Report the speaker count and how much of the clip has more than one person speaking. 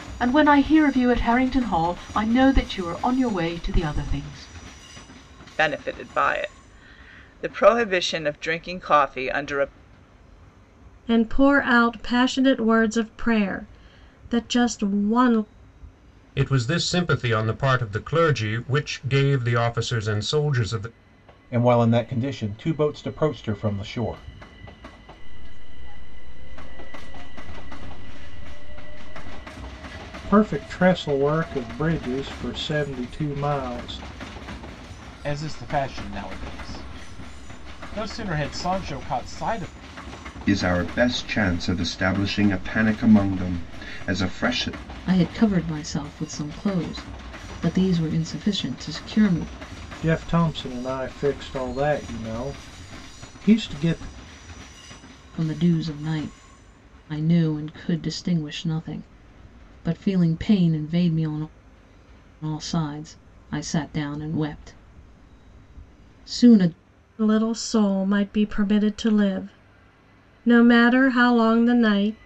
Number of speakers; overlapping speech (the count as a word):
ten, no overlap